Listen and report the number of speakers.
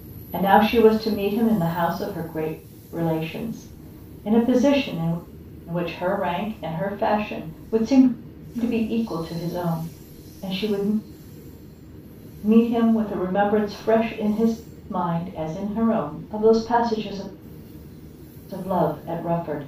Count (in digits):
1